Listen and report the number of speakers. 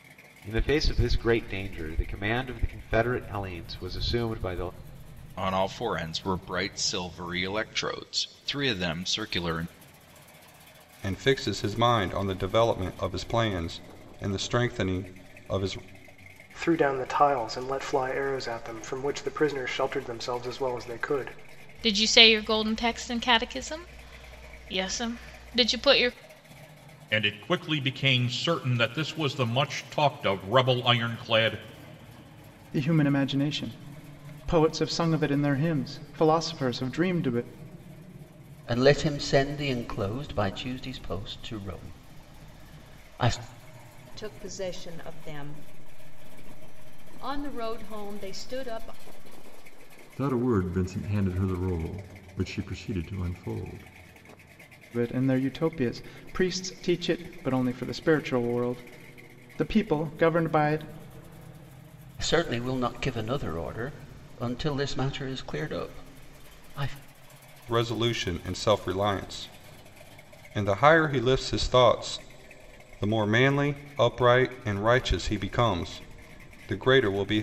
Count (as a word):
ten